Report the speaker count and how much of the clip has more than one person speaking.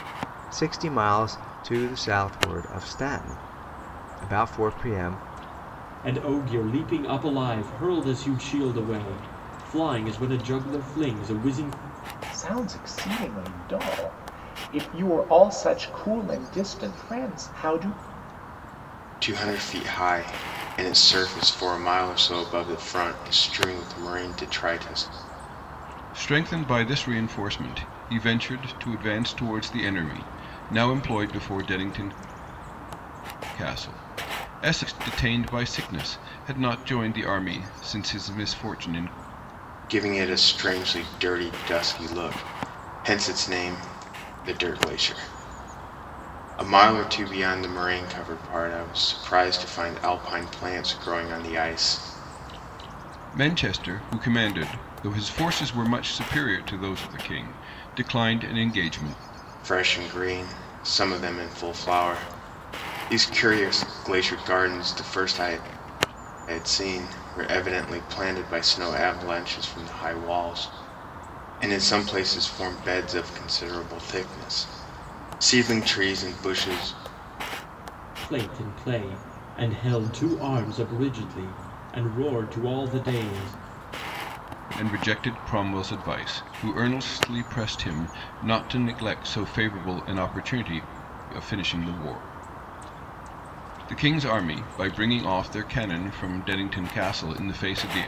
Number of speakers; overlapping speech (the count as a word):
five, no overlap